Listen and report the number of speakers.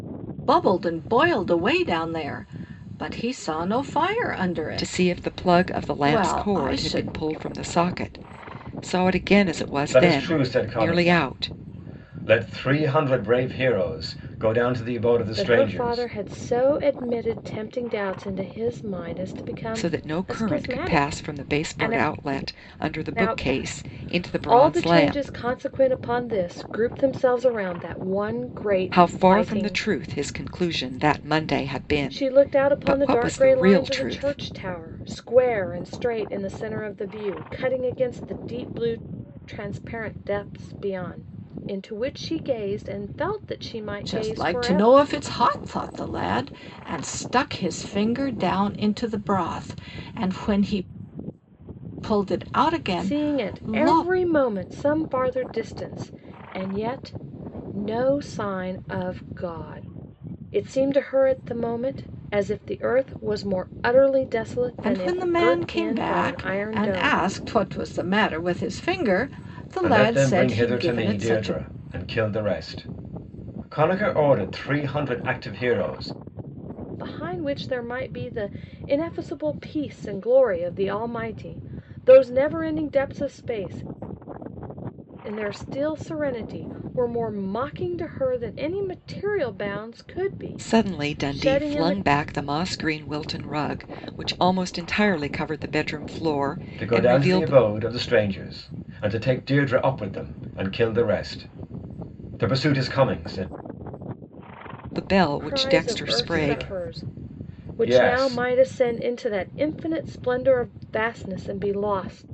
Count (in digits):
4